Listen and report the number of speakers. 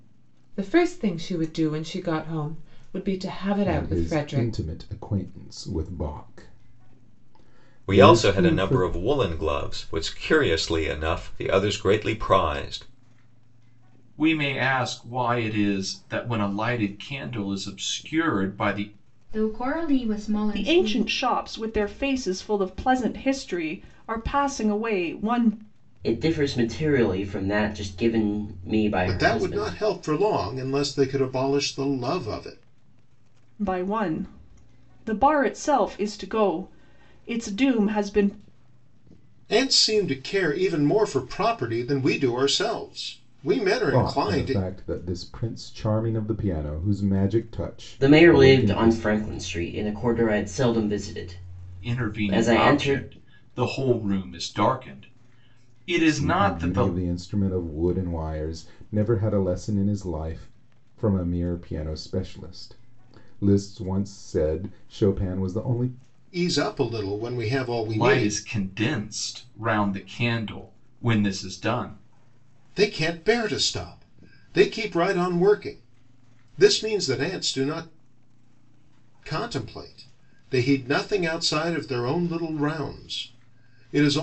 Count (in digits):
8